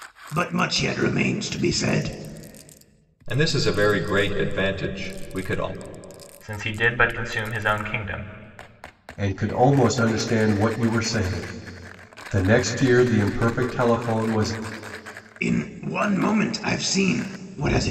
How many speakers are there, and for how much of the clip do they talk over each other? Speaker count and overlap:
4, no overlap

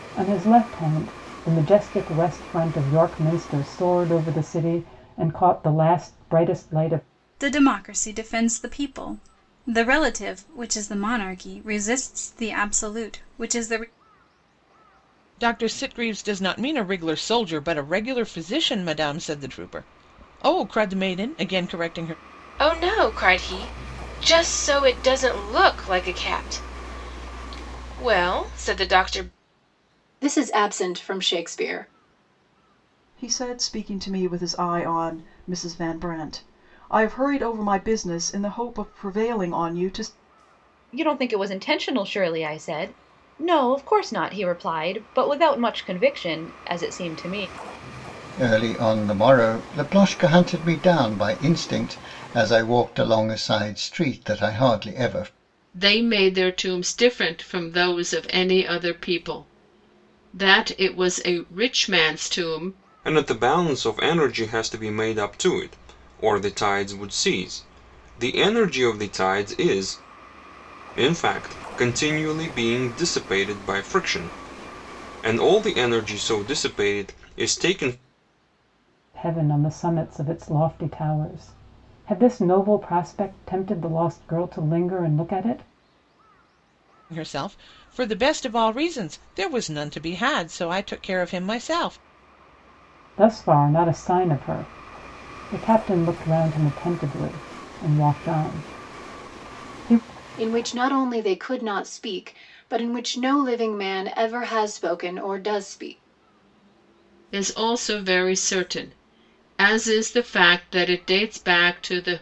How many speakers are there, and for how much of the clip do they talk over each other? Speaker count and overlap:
10, no overlap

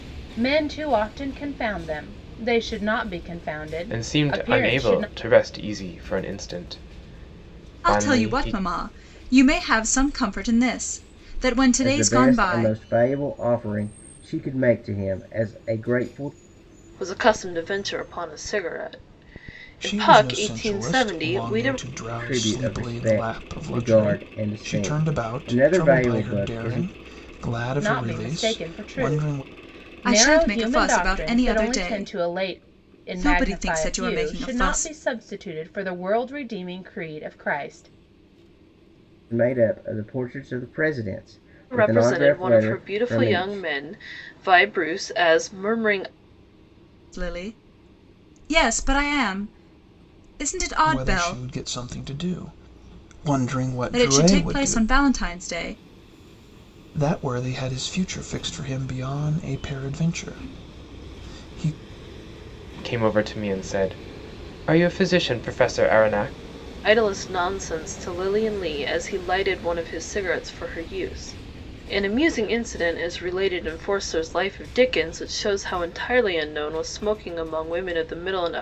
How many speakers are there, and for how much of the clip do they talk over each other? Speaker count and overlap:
6, about 24%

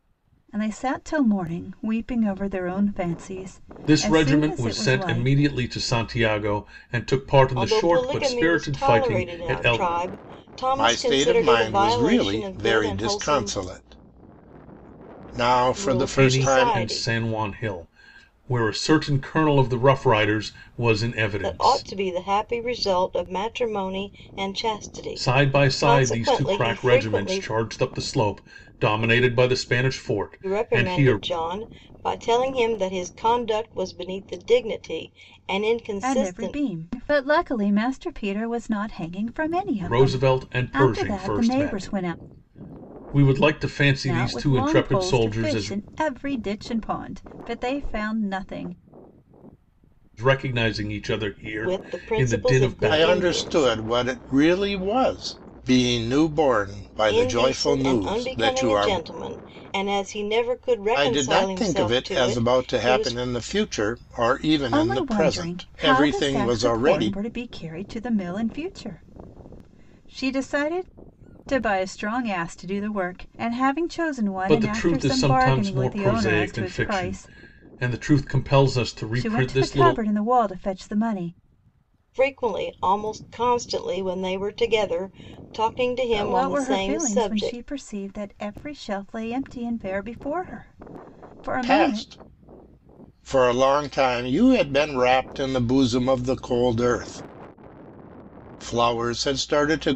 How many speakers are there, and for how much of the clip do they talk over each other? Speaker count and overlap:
4, about 31%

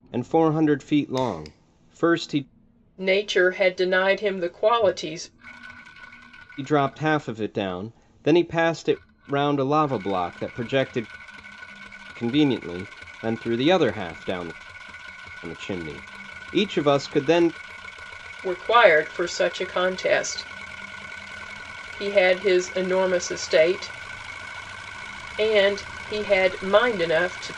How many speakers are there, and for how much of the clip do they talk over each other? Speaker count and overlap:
2, no overlap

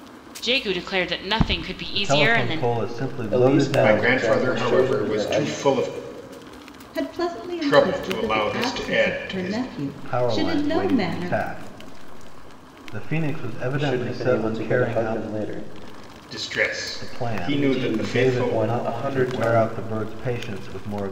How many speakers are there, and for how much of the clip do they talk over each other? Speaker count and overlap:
5, about 52%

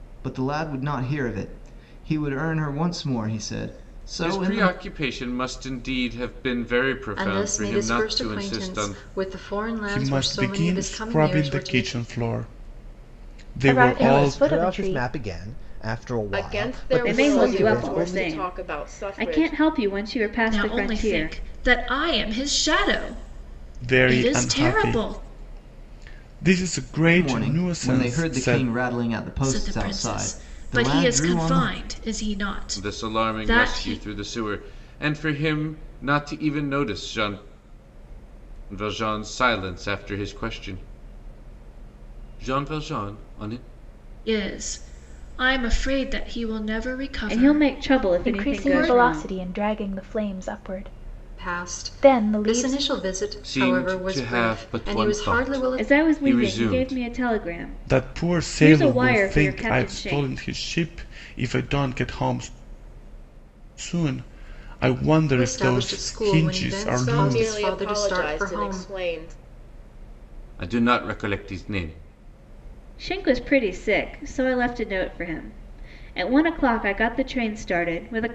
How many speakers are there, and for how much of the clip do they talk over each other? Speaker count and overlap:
9, about 38%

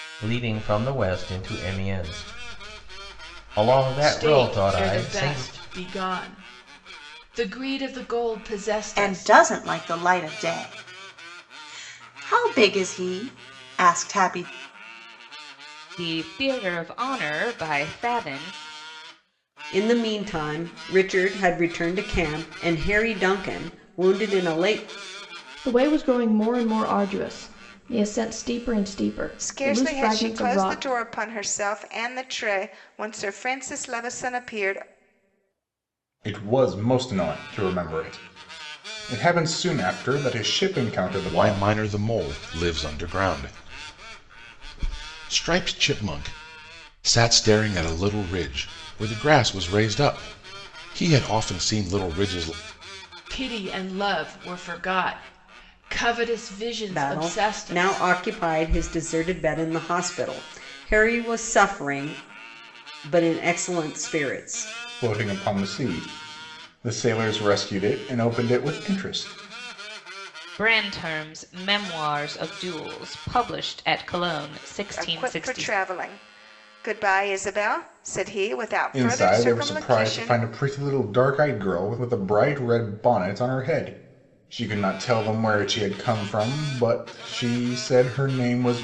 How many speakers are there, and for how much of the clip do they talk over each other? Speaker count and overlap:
9, about 8%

